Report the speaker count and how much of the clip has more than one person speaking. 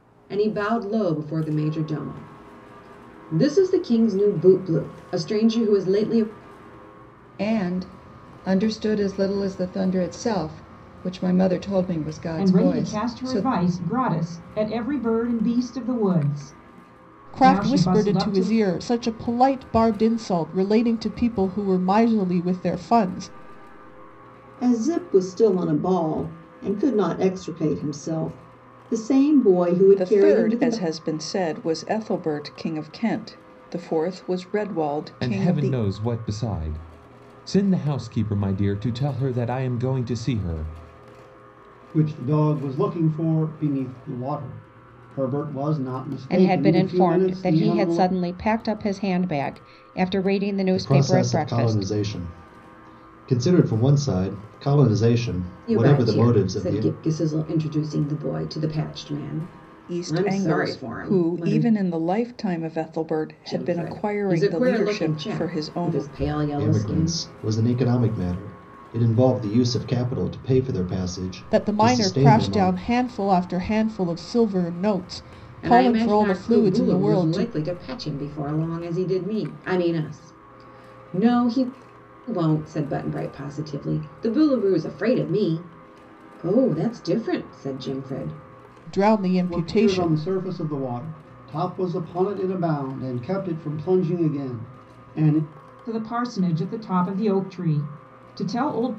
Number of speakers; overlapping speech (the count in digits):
10, about 17%